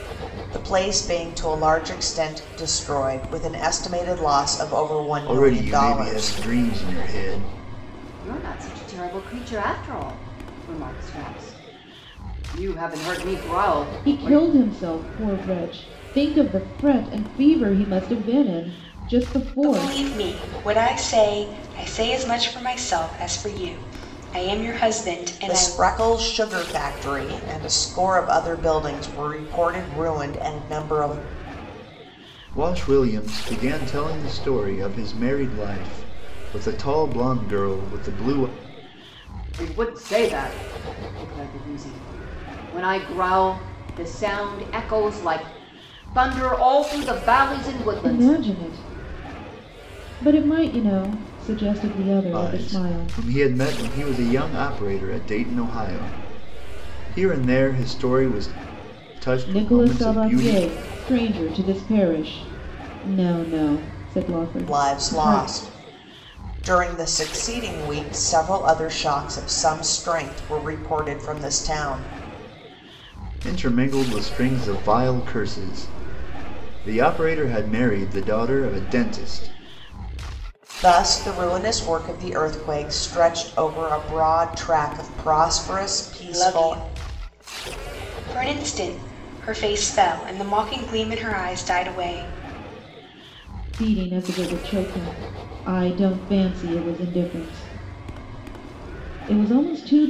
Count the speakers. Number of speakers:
five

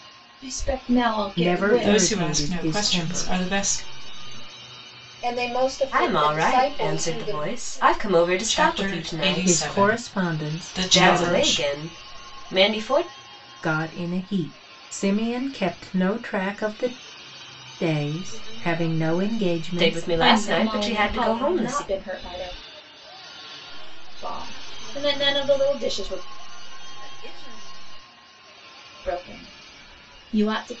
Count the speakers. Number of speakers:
six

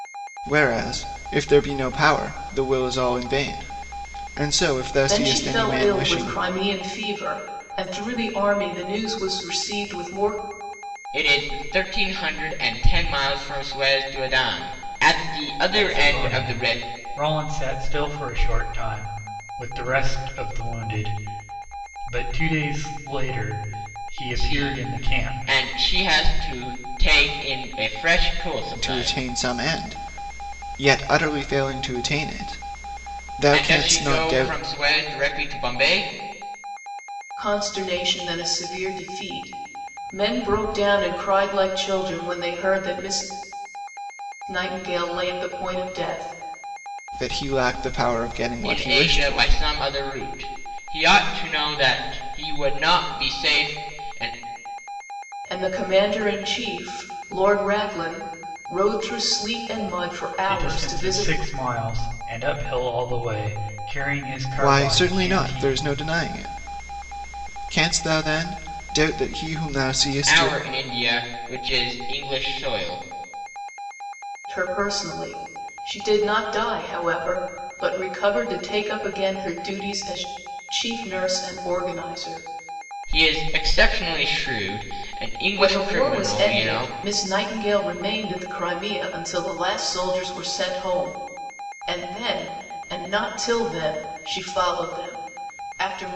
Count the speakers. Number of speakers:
four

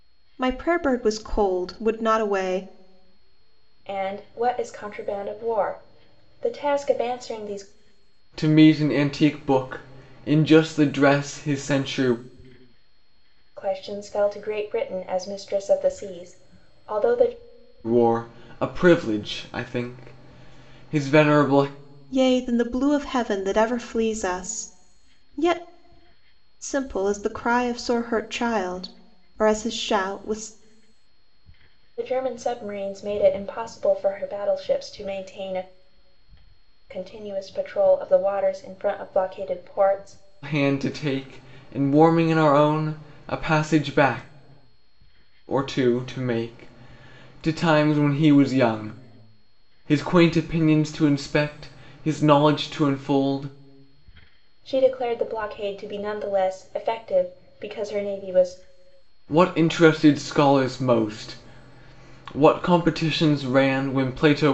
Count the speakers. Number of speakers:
three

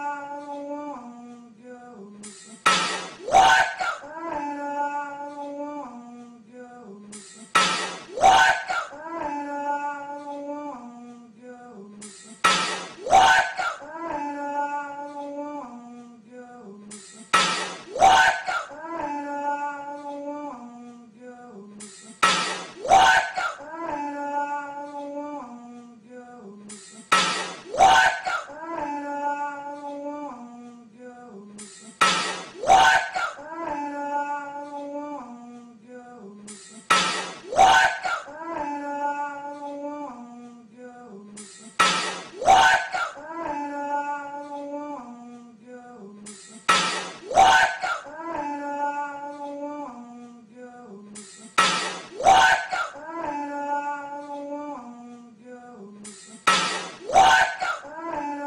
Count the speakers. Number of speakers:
zero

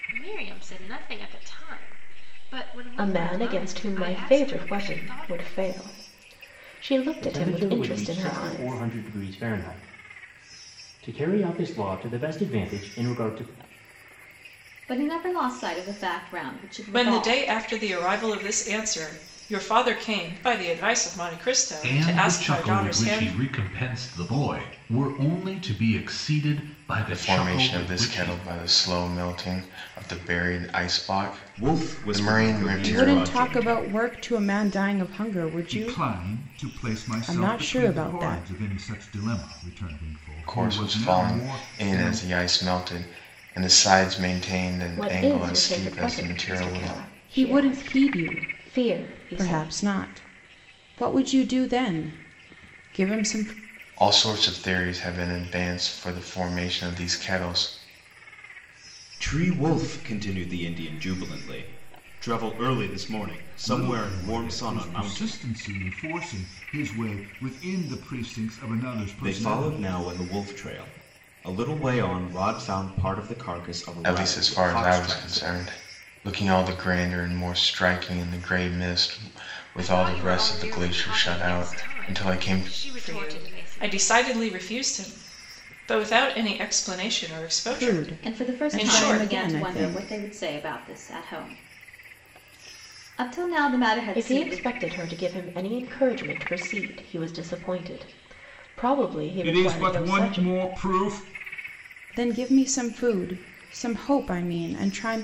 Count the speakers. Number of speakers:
ten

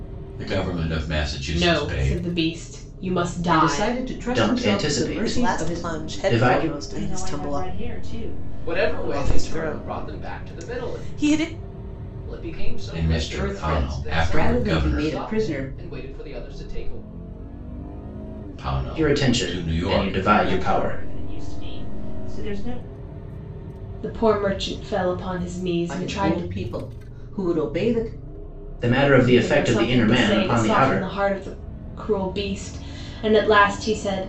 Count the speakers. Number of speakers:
seven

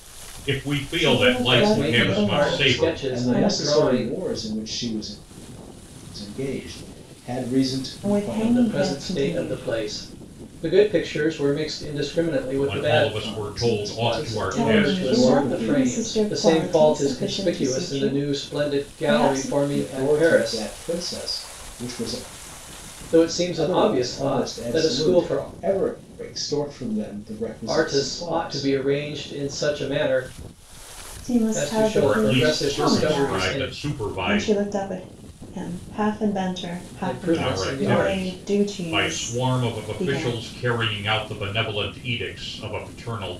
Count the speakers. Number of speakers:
four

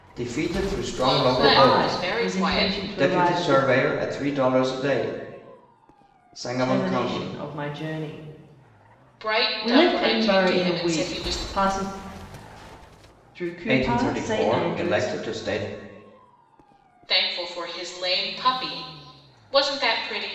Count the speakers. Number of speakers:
three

